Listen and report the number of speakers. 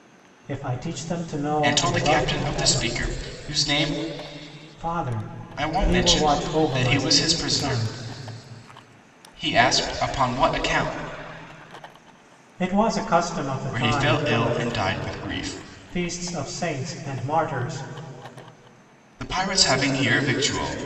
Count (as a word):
two